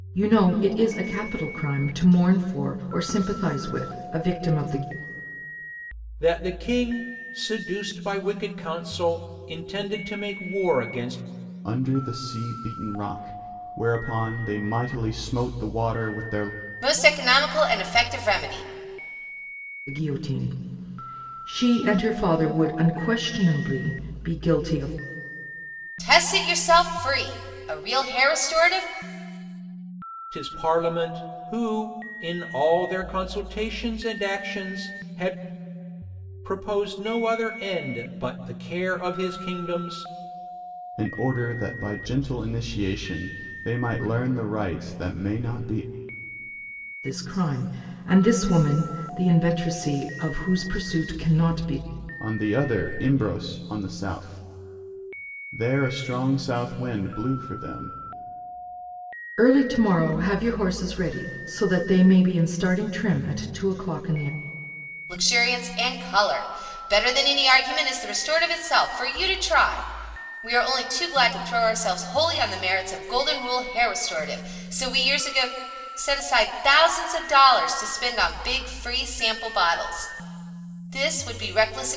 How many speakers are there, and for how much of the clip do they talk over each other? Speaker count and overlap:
four, no overlap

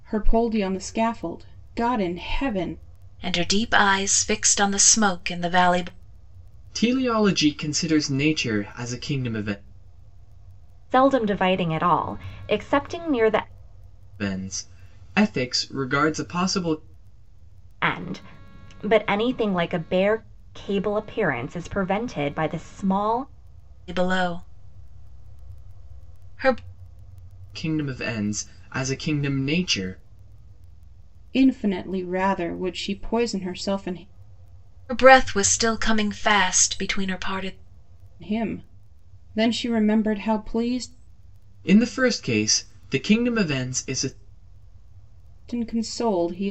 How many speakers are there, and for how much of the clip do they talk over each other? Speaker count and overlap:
four, no overlap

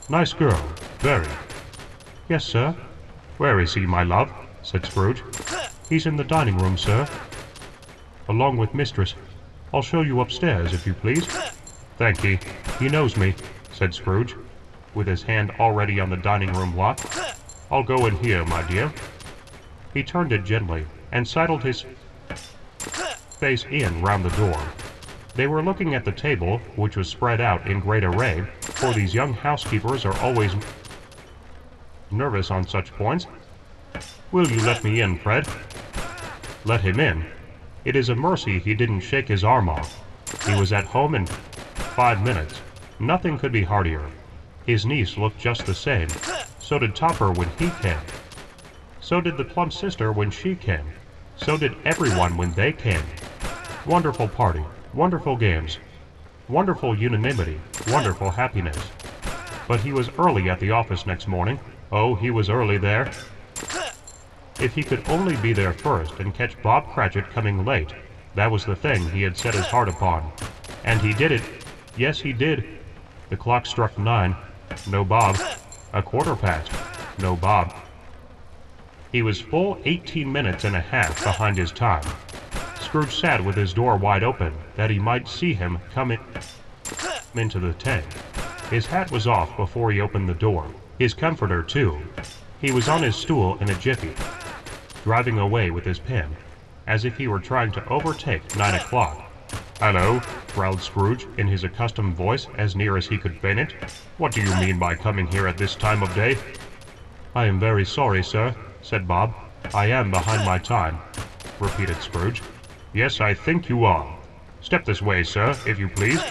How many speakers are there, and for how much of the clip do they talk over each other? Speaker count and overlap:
one, no overlap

